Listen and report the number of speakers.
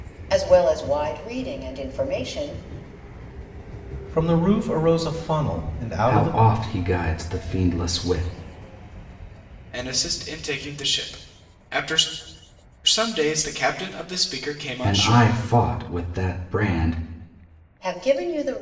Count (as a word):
four